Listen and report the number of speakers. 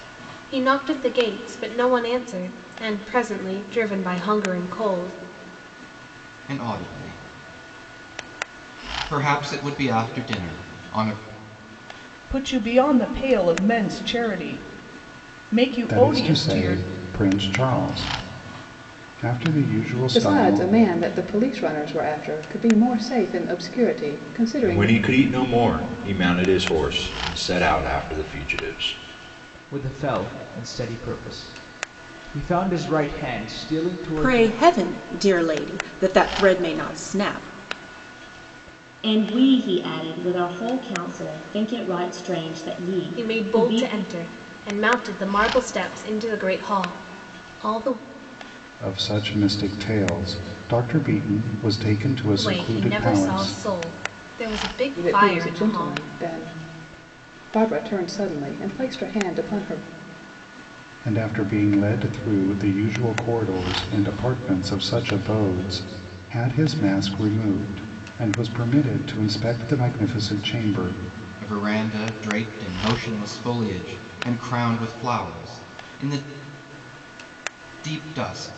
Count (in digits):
9